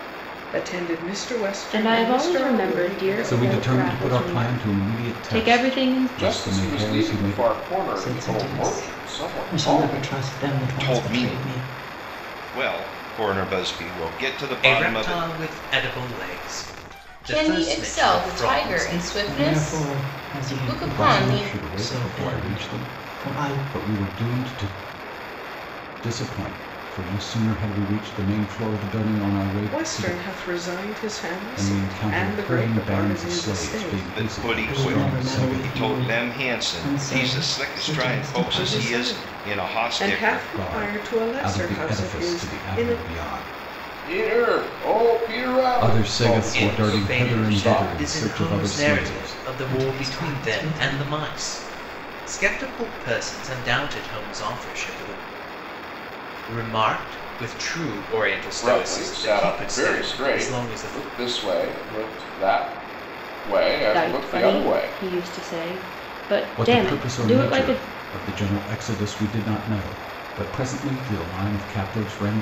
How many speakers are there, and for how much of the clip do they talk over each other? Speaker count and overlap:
8, about 52%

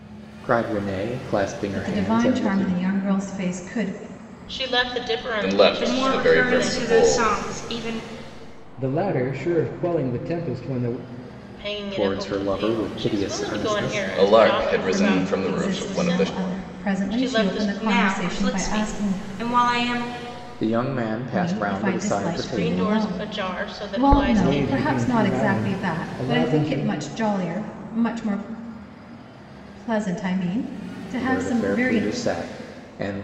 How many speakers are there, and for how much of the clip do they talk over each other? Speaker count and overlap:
6, about 48%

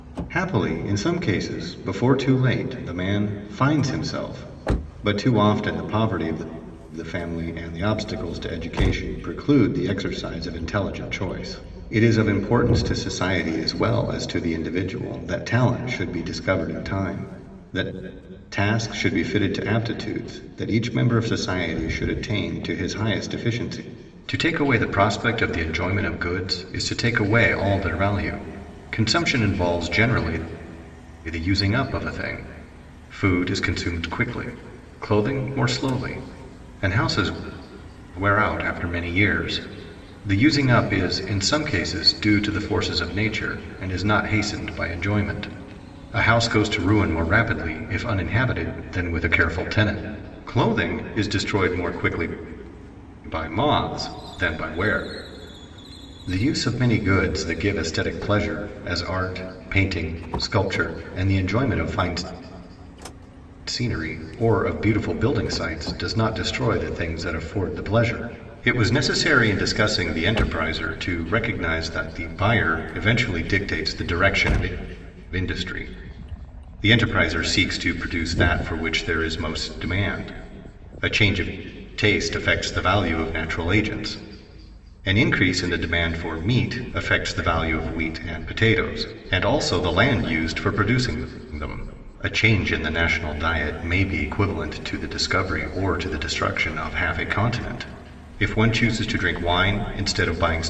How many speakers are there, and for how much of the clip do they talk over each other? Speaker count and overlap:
1, no overlap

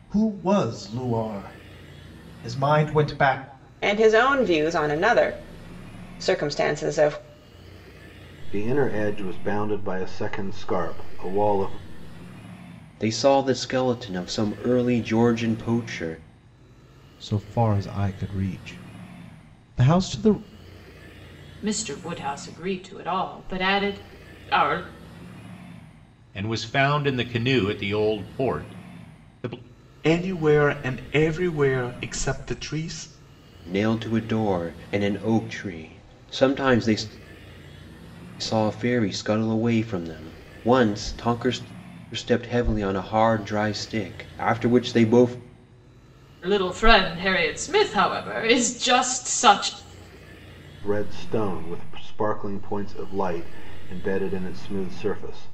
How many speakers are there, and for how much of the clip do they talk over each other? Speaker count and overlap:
8, no overlap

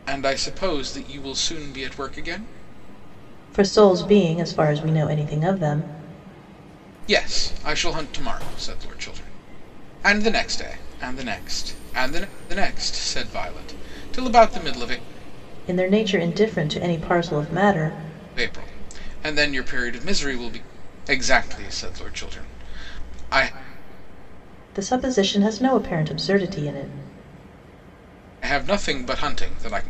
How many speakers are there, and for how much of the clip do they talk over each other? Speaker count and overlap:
2, no overlap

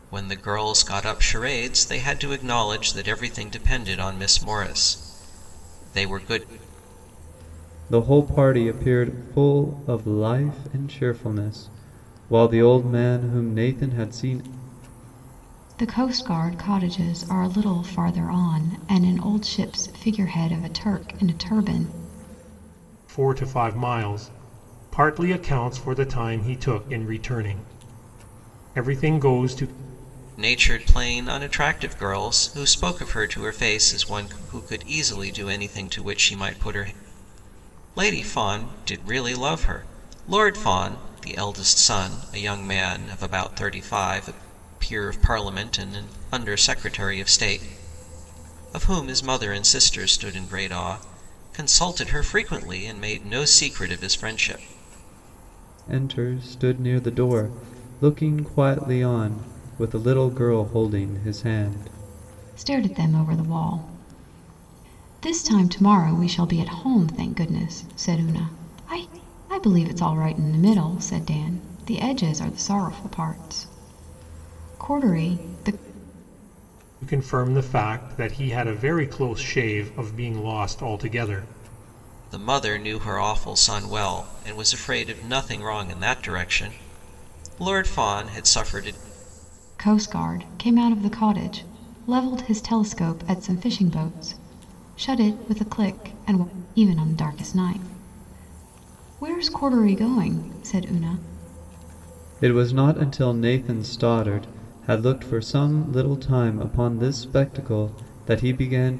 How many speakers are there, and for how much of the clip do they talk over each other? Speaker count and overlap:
4, no overlap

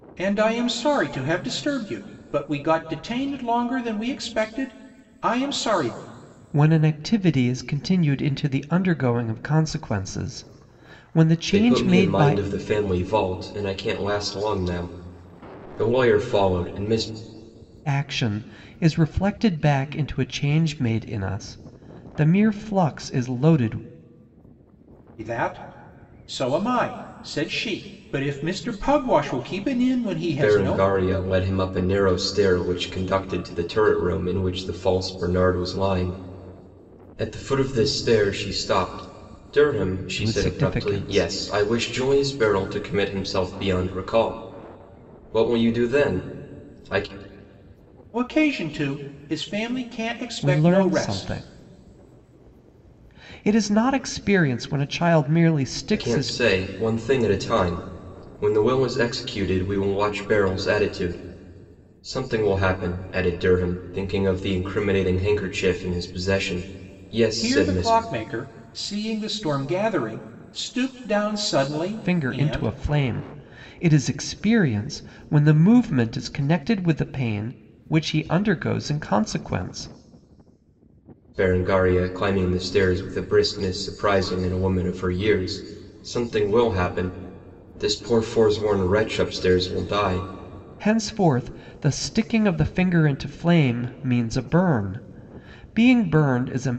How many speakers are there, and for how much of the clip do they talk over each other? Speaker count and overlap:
3, about 6%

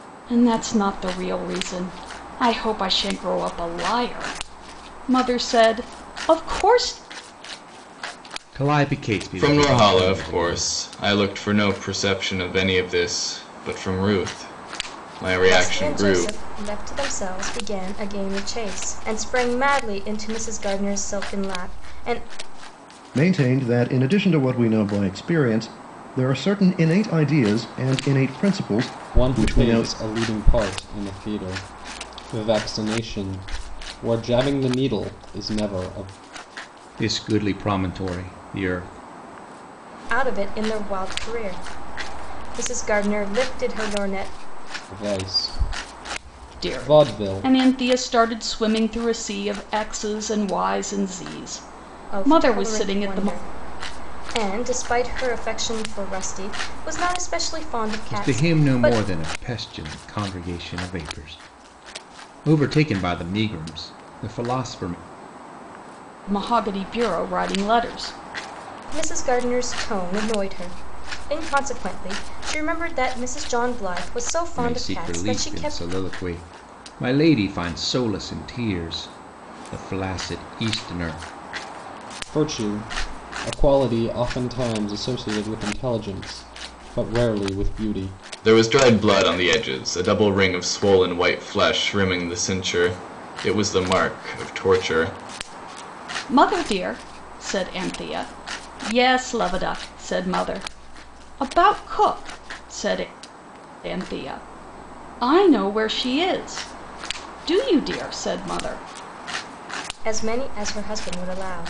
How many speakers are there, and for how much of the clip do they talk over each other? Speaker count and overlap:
6, about 7%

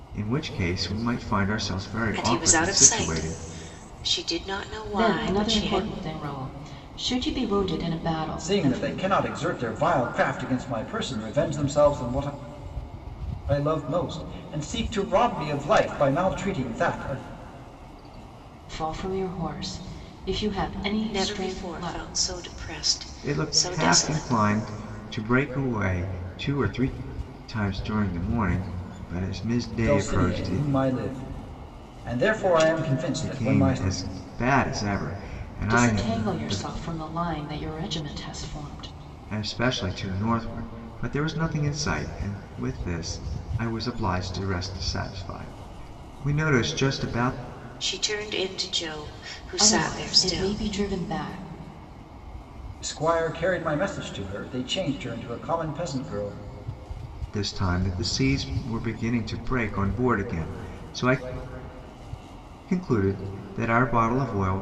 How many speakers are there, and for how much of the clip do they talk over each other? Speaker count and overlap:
4, about 14%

